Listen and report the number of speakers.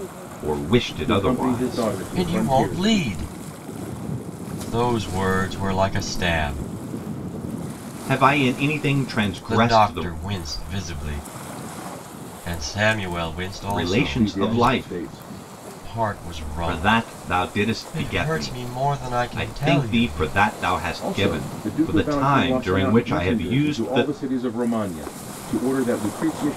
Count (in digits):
3